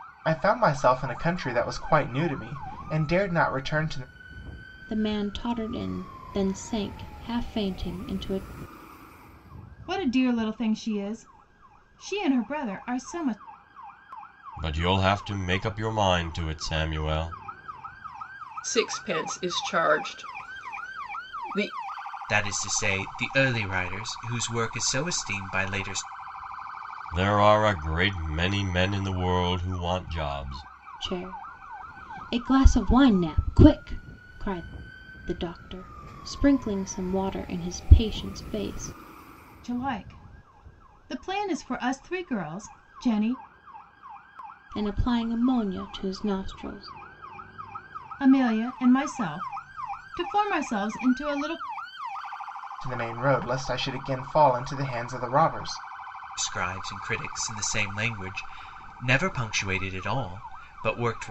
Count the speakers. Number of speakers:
six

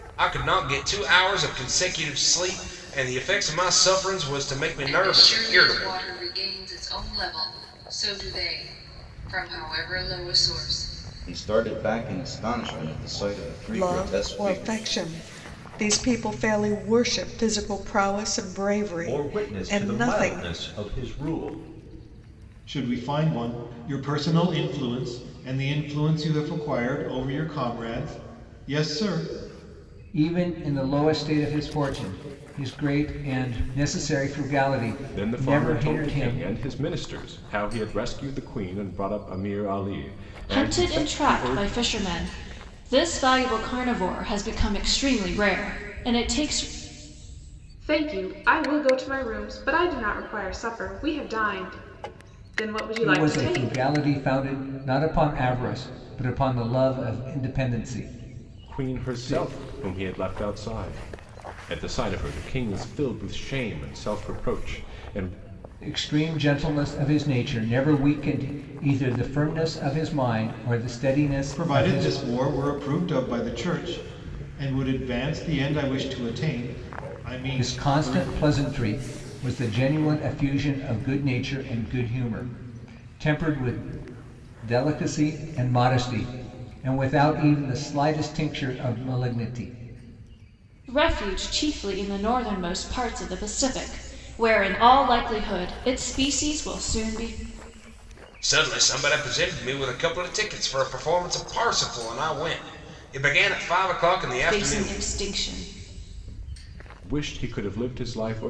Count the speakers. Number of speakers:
ten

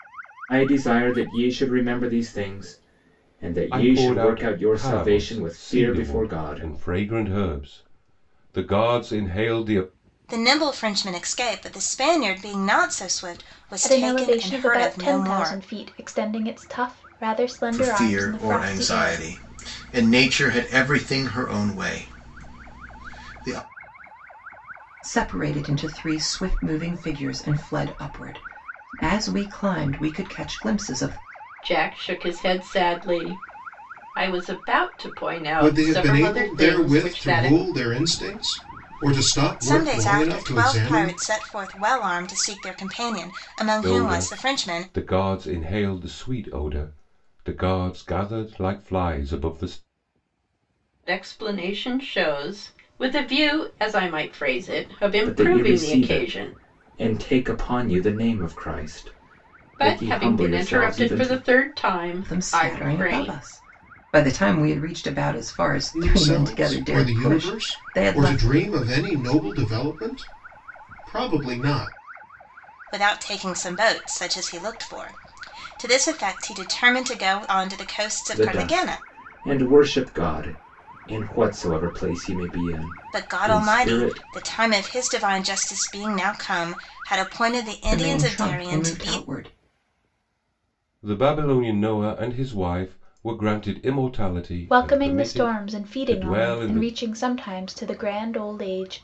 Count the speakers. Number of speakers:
eight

